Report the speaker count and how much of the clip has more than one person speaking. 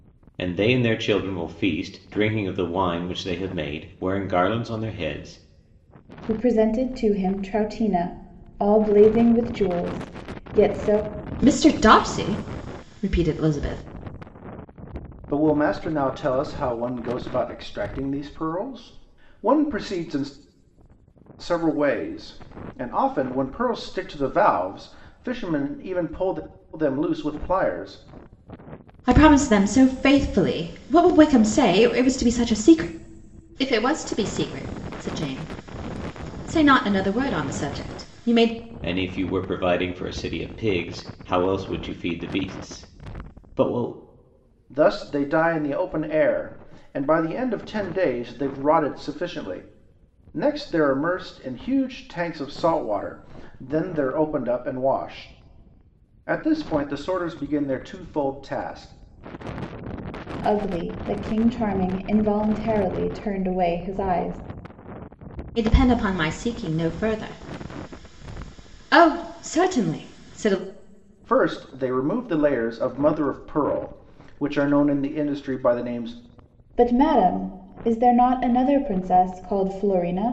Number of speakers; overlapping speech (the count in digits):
4, no overlap